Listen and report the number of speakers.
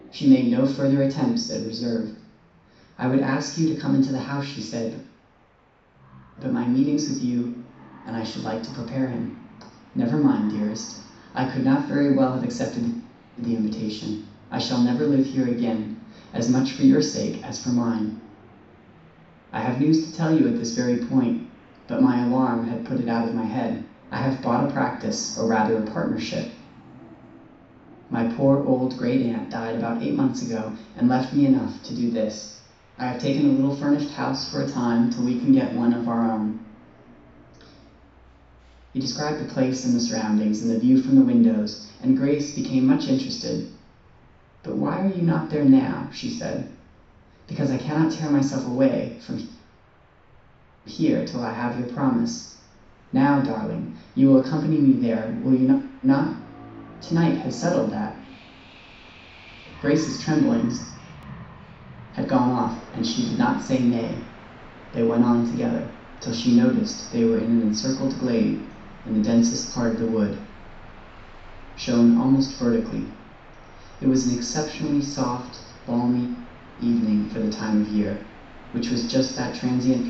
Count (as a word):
one